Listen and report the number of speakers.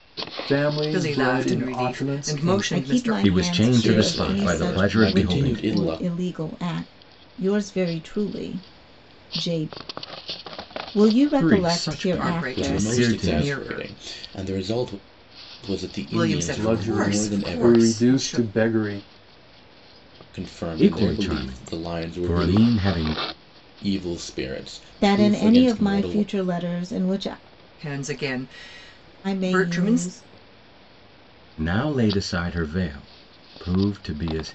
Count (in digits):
5